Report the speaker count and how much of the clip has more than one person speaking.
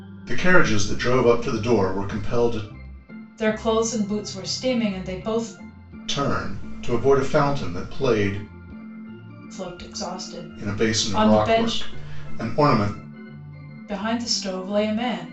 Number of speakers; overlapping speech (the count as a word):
two, about 9%